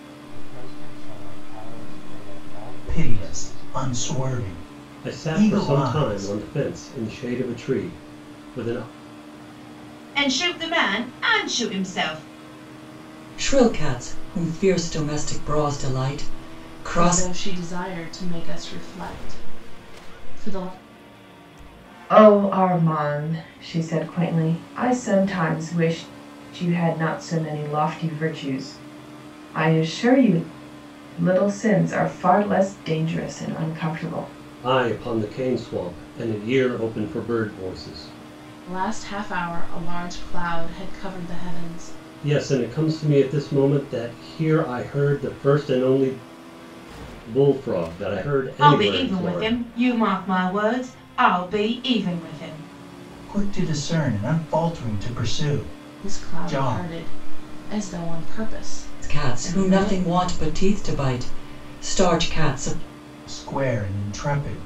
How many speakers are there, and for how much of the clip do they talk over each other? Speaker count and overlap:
7, about 9%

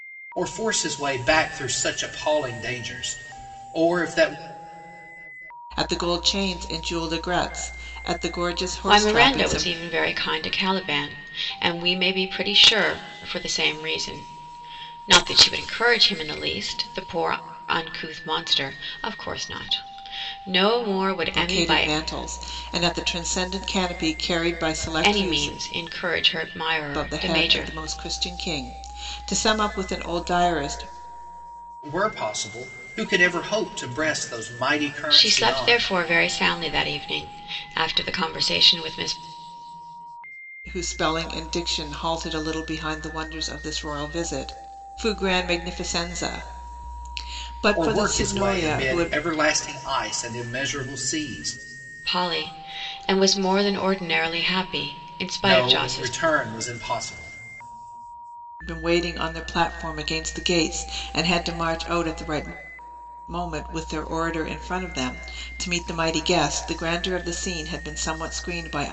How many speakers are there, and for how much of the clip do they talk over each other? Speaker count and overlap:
3, about 9%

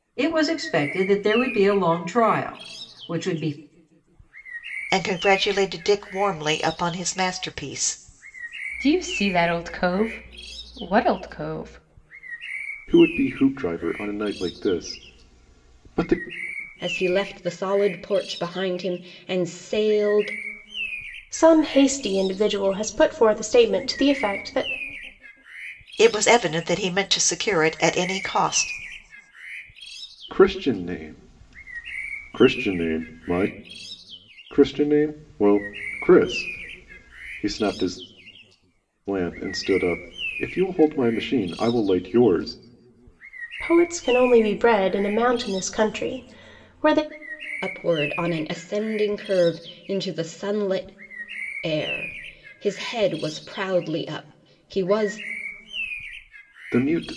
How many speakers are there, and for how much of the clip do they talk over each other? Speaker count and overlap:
6, no overlap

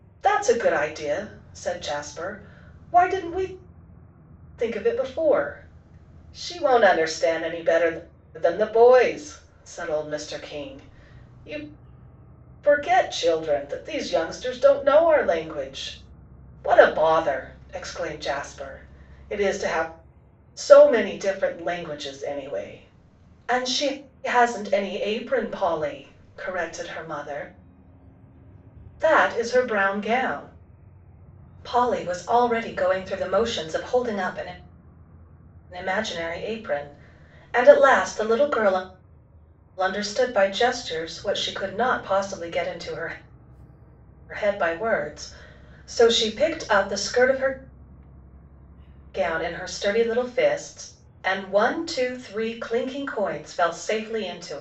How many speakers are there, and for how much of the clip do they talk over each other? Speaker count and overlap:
1, no overlap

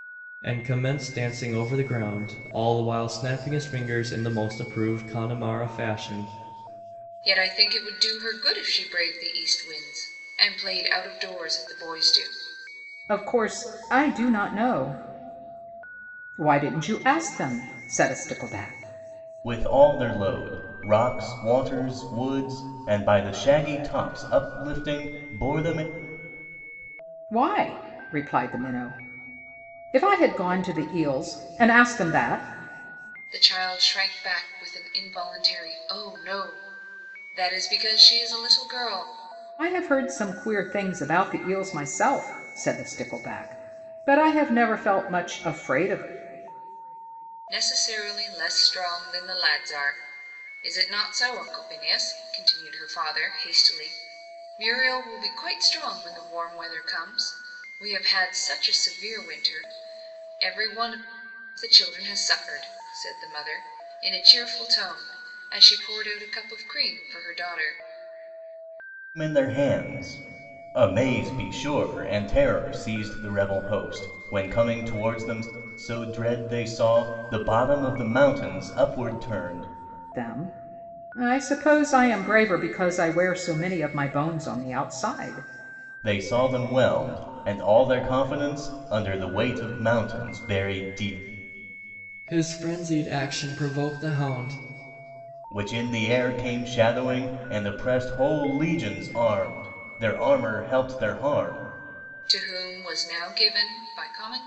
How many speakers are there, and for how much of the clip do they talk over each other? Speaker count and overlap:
4, no overlap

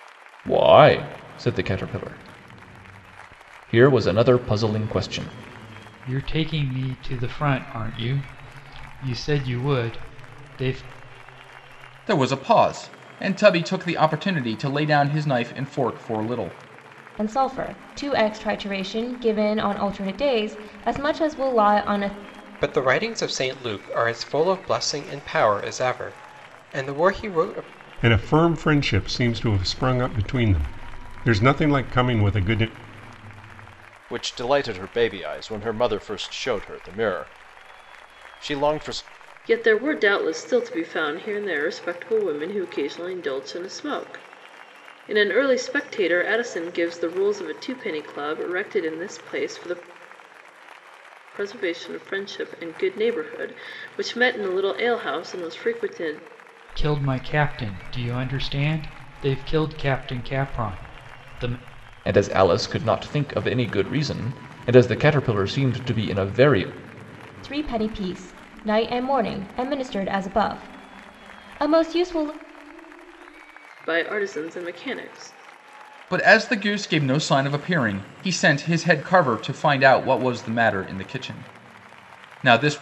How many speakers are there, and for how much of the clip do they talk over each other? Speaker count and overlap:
8, no overlap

